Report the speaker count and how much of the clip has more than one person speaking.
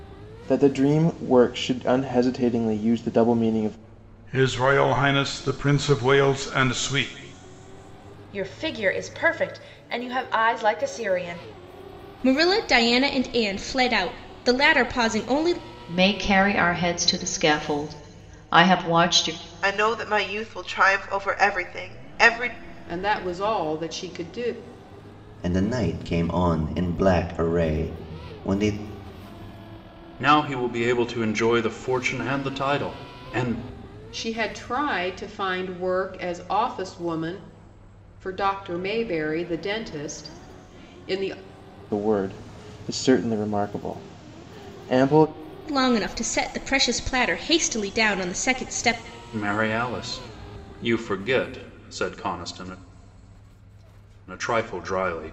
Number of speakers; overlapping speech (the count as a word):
nine, no overlap